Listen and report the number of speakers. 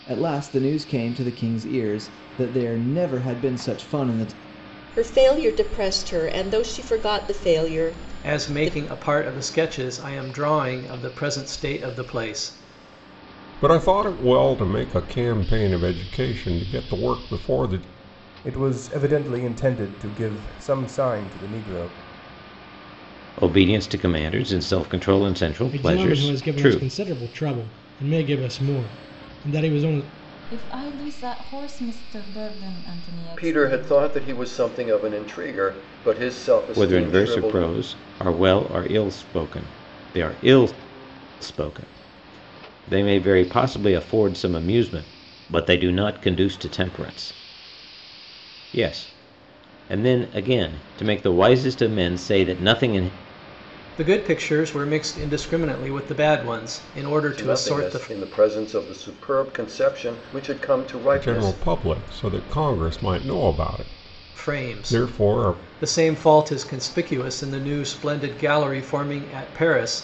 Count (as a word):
nine